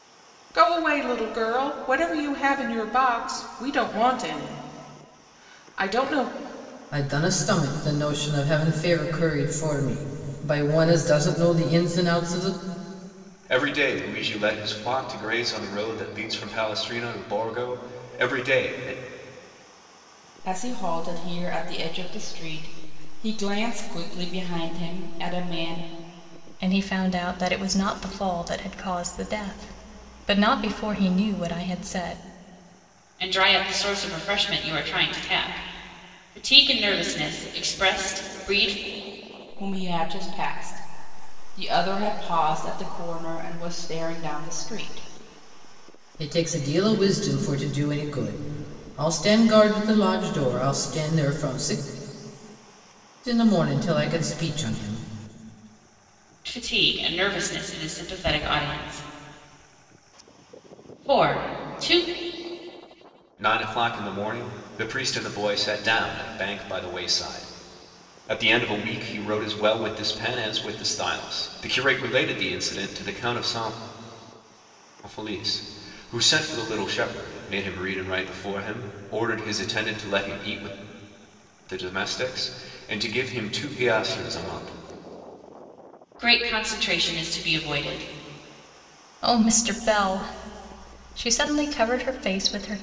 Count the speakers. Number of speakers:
six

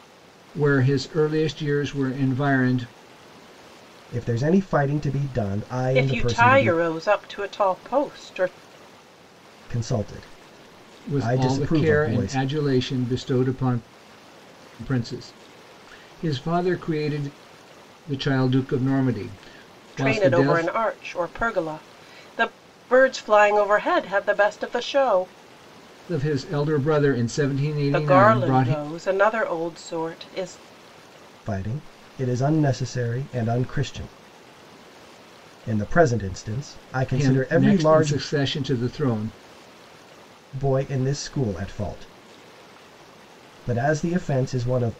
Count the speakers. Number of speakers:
three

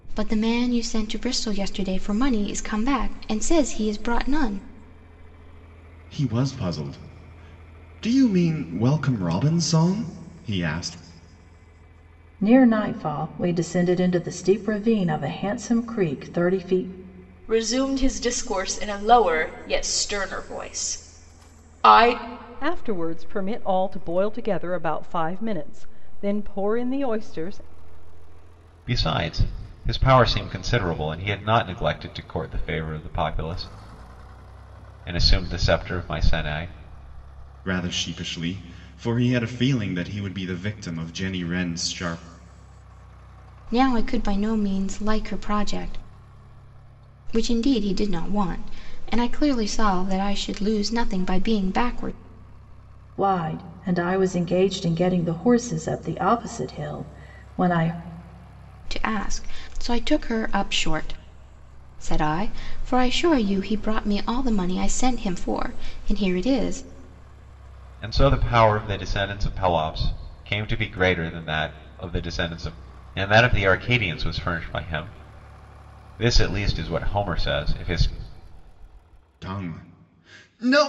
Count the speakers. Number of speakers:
six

